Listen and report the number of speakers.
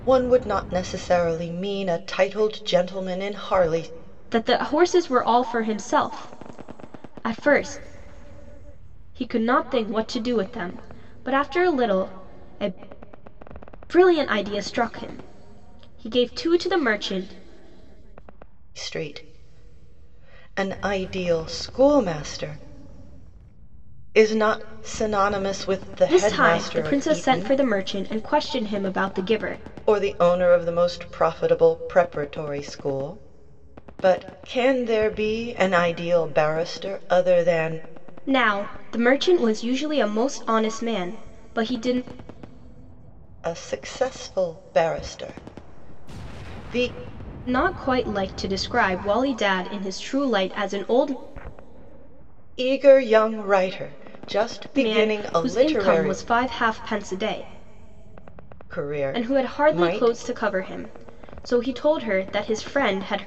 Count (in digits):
2